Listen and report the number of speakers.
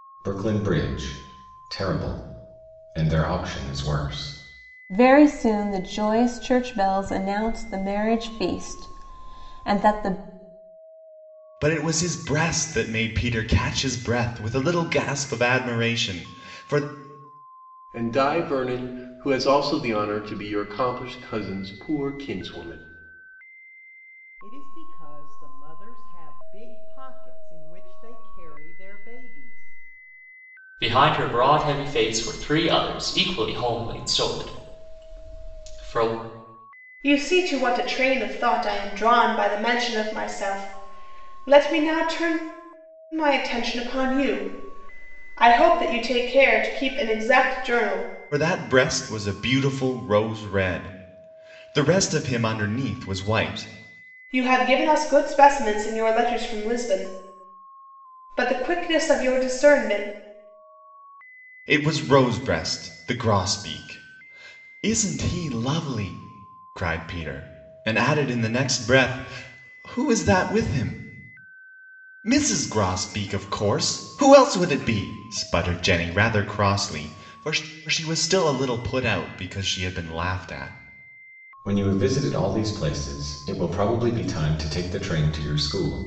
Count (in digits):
7